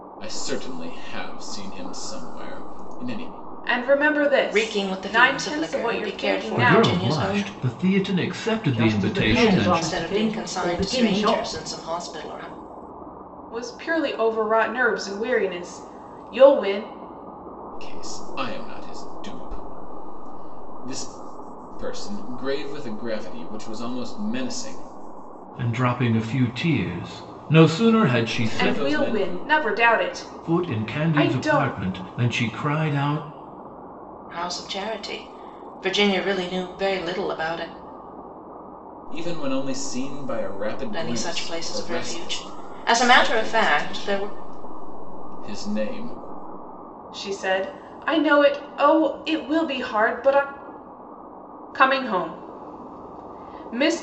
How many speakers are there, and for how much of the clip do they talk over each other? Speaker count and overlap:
five, about 21%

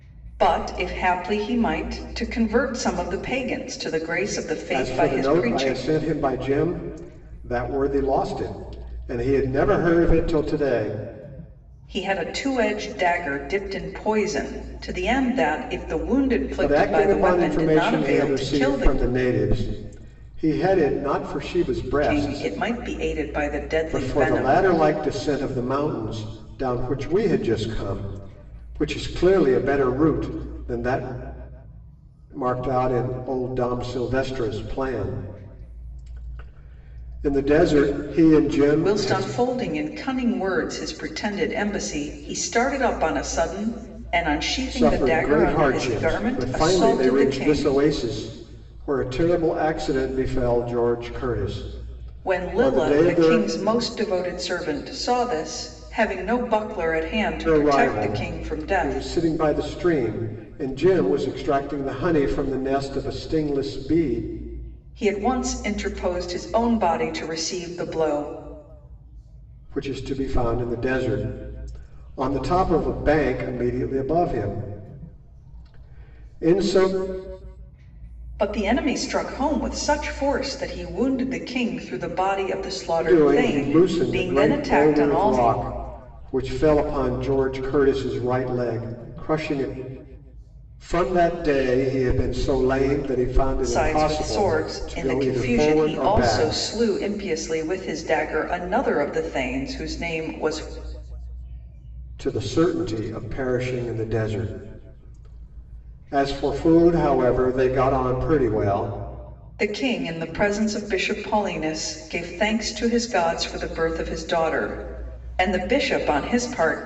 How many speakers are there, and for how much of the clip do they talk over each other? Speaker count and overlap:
two, about 14%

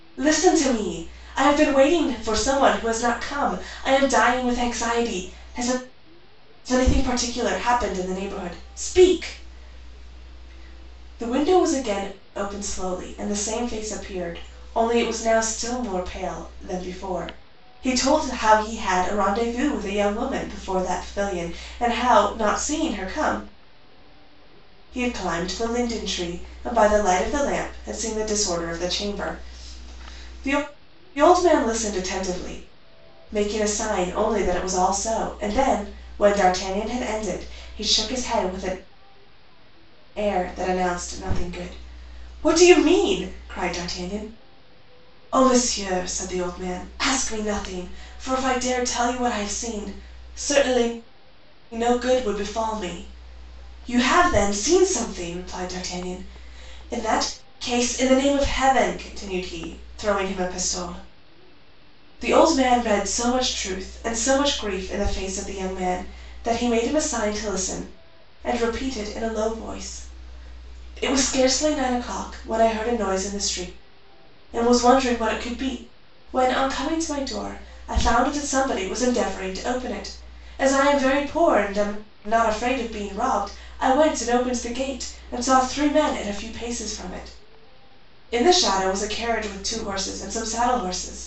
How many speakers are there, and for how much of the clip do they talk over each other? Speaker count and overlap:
one, no overlap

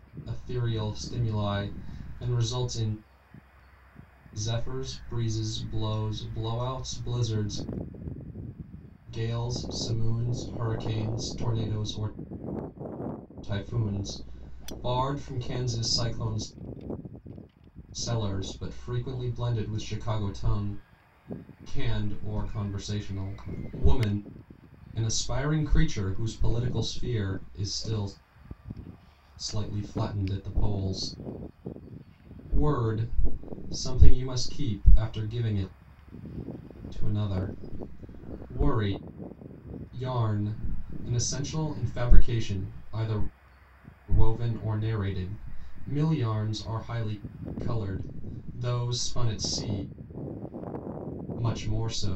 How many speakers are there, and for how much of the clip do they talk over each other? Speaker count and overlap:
one, no overlap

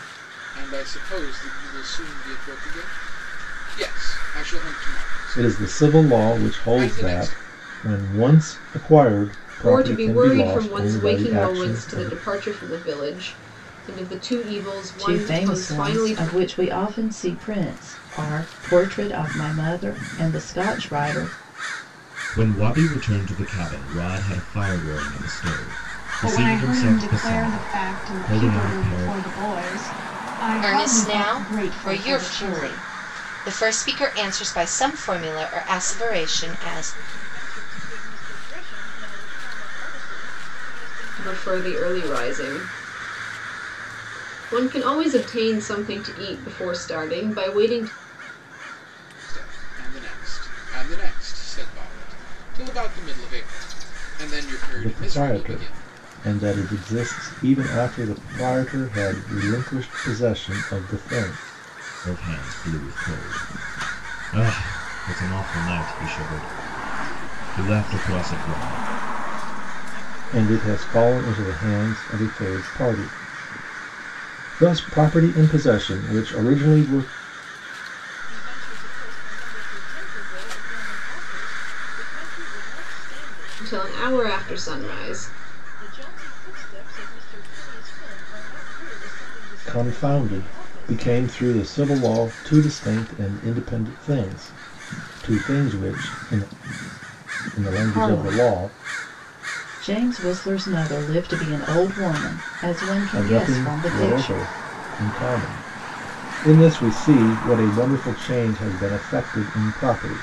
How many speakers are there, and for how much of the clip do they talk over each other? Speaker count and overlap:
eight, about 21%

